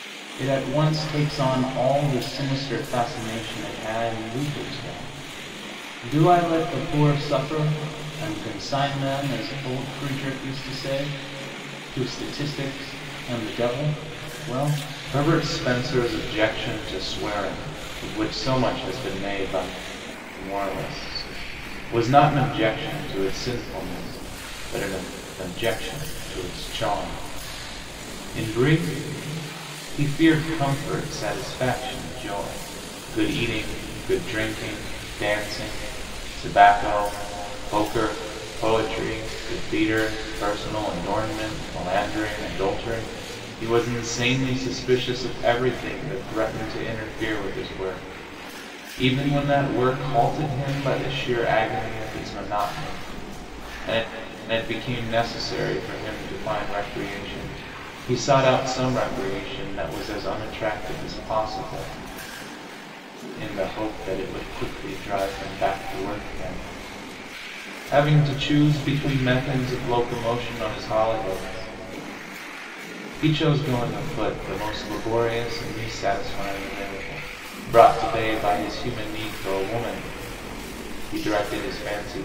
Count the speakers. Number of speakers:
1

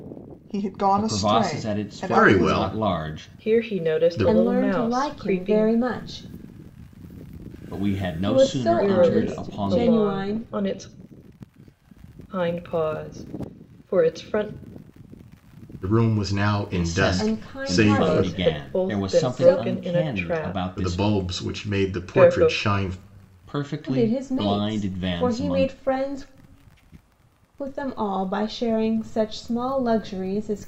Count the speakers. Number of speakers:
5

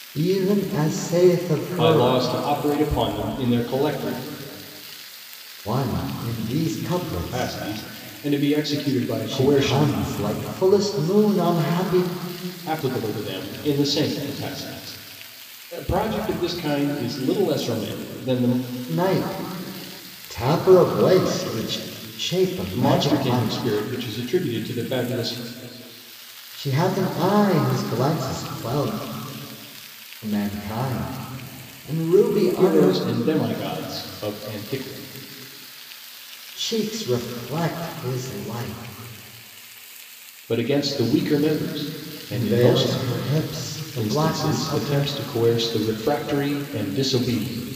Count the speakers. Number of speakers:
2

